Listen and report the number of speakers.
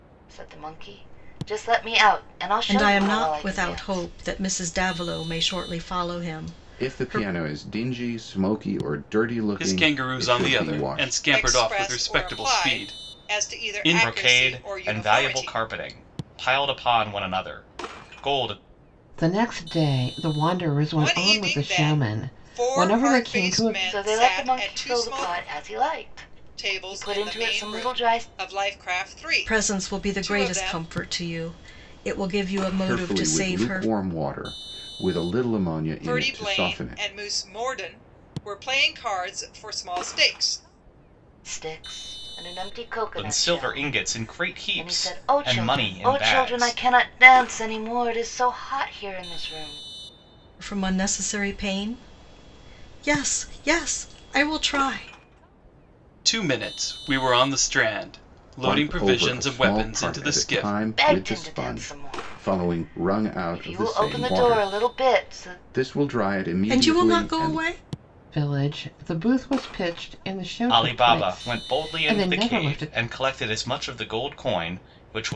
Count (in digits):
7